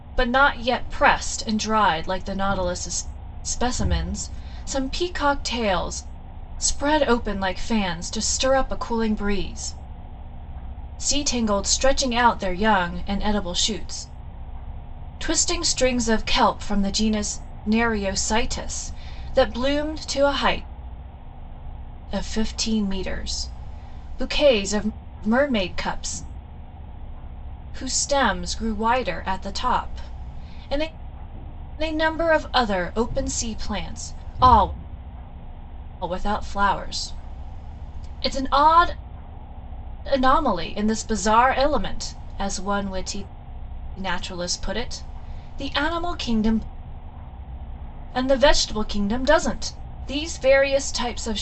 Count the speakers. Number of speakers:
one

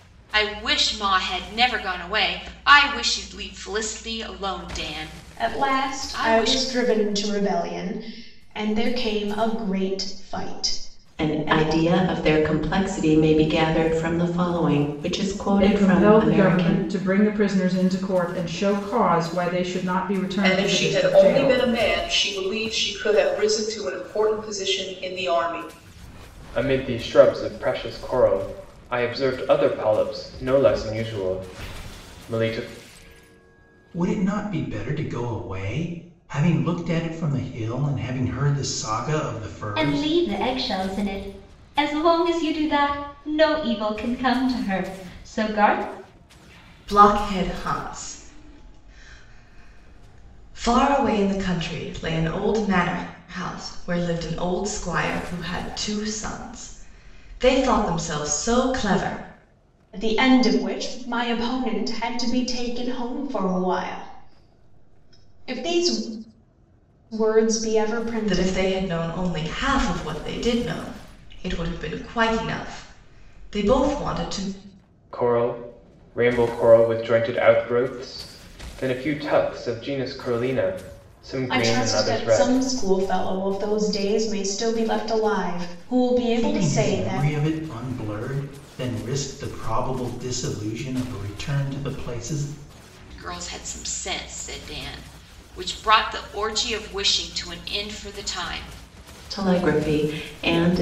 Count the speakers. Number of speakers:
nine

